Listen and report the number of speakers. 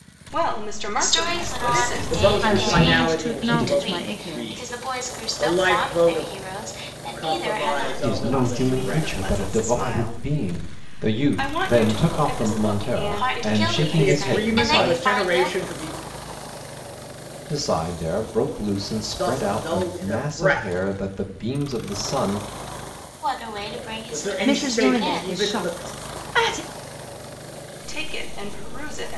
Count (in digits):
5